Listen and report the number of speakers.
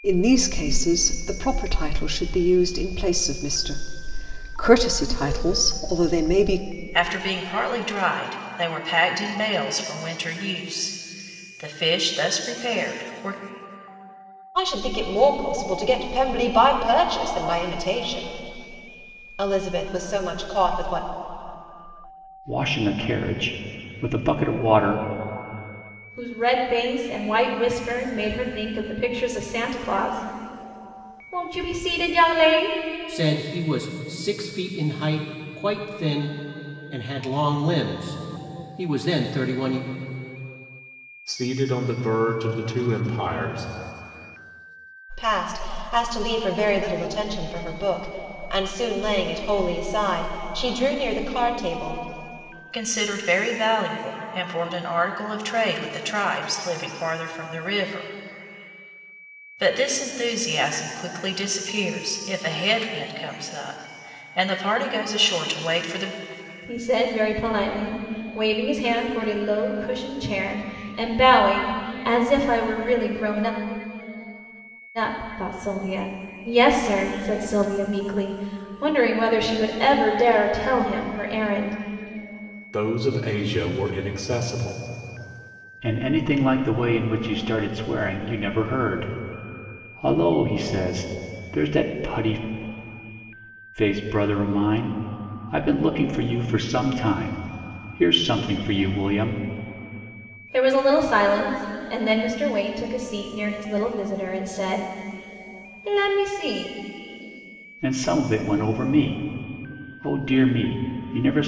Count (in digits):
7